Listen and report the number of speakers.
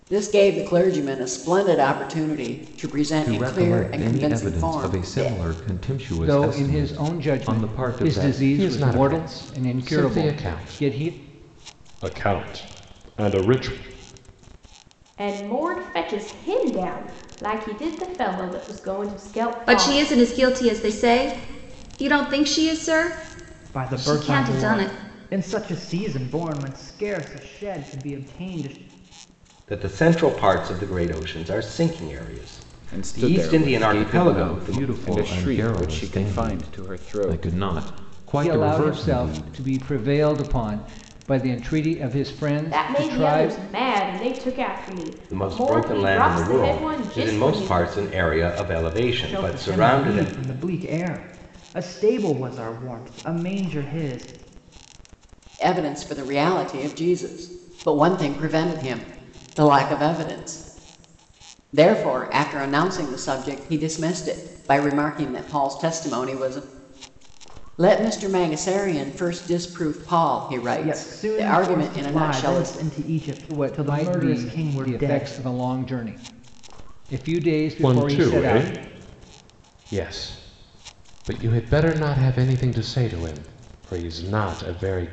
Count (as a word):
nine